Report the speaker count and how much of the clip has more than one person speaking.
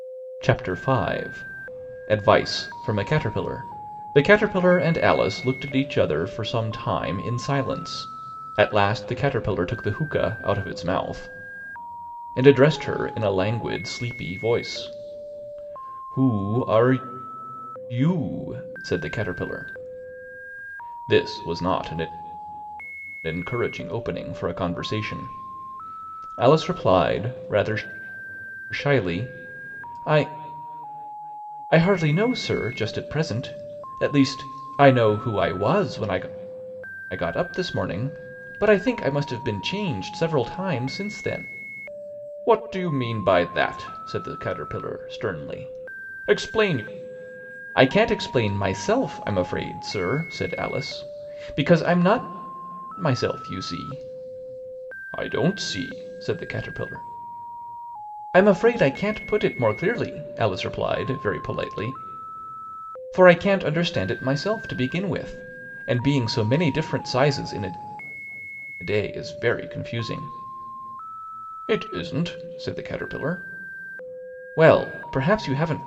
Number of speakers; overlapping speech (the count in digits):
1, no overlap